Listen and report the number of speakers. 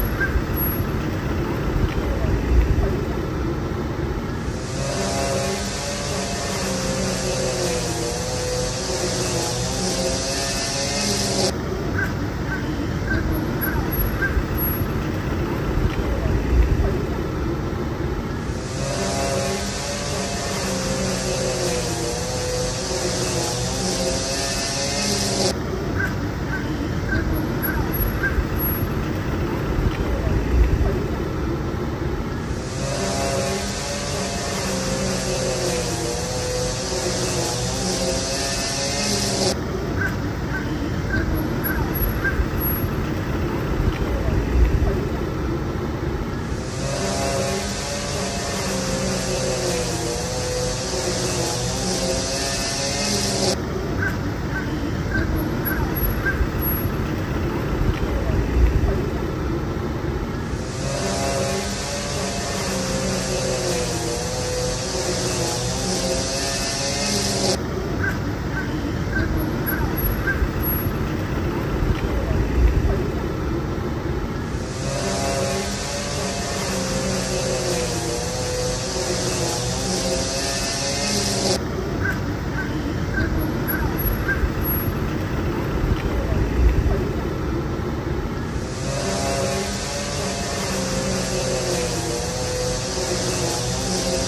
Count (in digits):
0